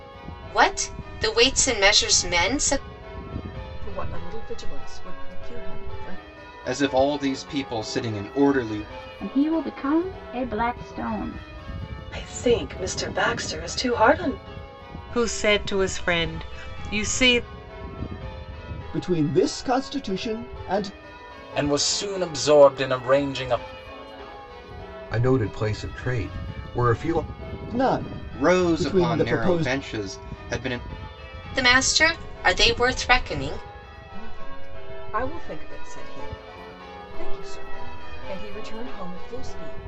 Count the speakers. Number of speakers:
nine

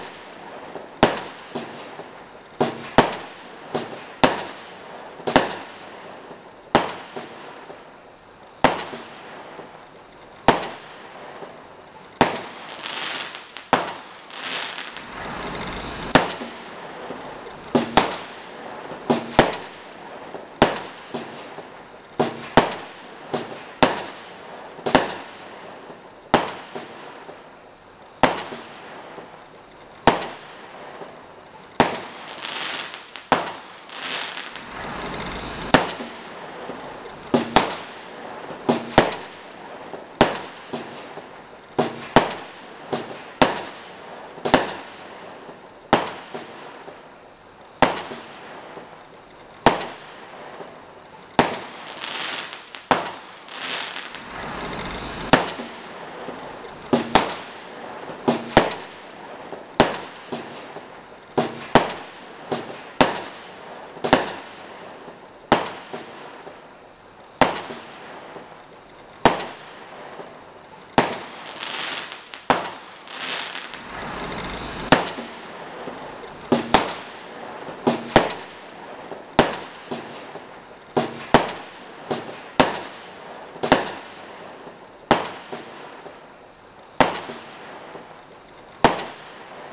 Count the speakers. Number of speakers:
zero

